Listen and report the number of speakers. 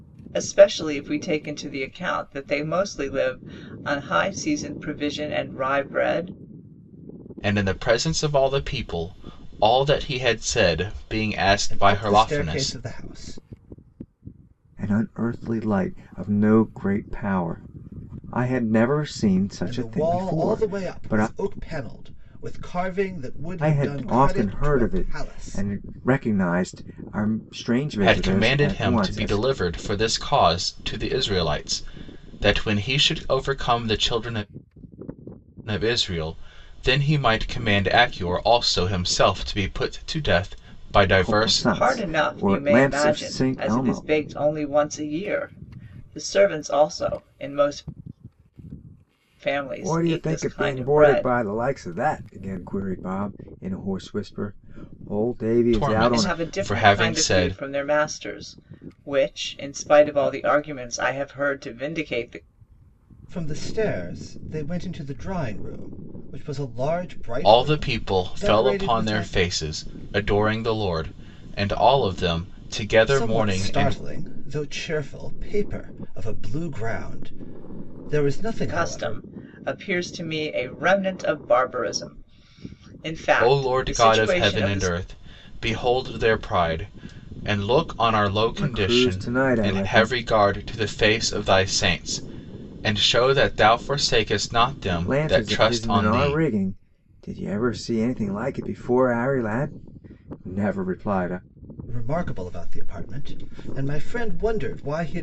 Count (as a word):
four